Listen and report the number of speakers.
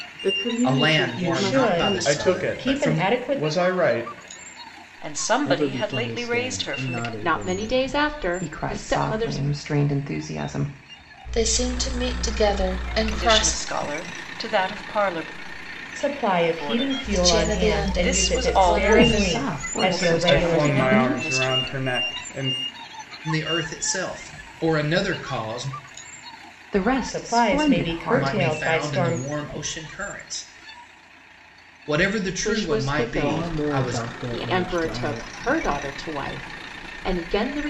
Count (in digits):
9